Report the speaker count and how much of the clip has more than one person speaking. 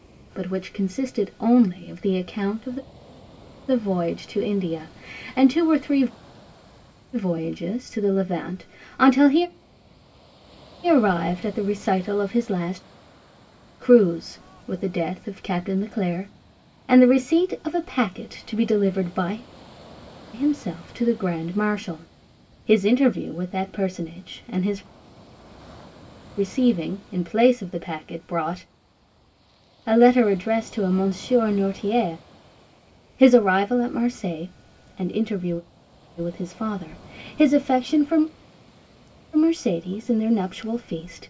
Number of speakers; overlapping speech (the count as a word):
one, no overlap